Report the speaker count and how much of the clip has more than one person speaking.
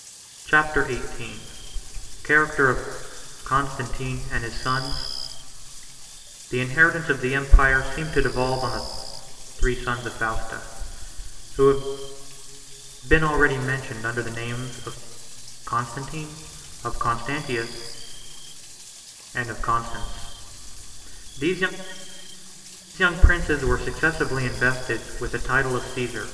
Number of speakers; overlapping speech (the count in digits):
1, no overlap